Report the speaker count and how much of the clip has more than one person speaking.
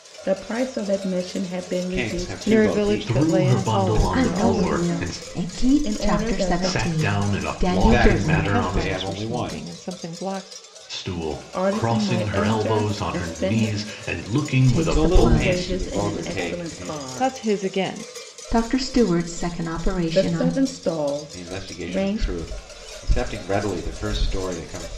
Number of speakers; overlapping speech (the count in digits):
5, about 58%